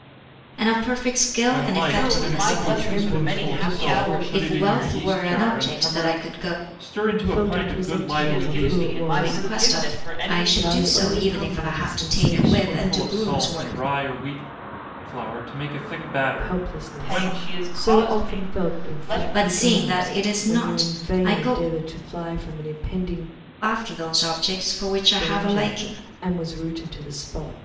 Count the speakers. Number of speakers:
four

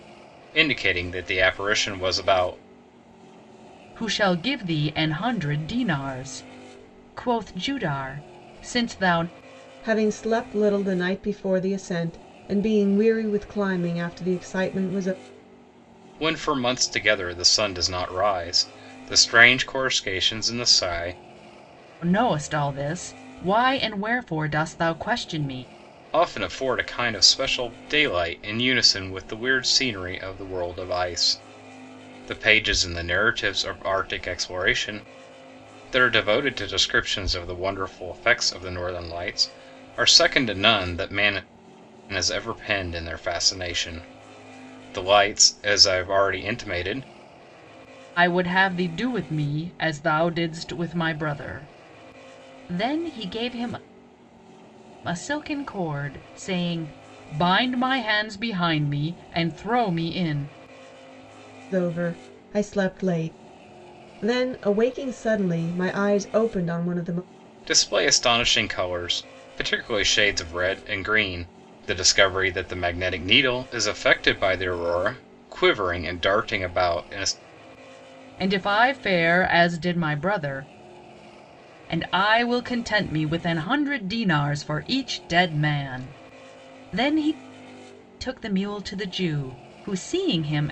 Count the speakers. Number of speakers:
three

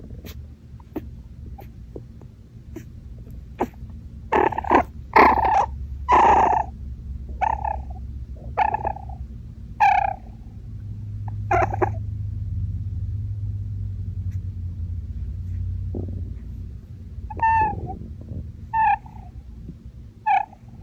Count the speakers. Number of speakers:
zero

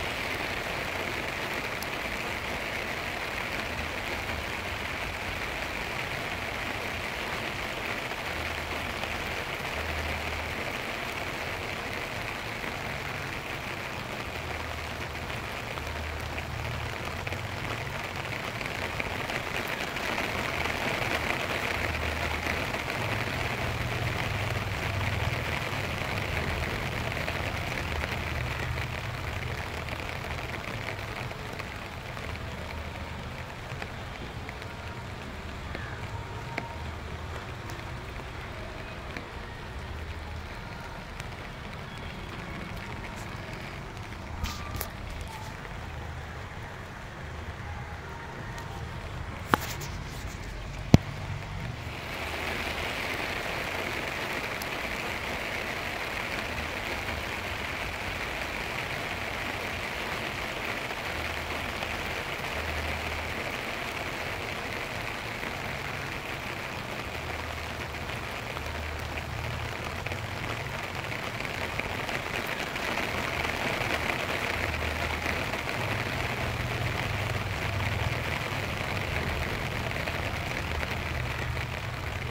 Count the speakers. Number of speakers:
zero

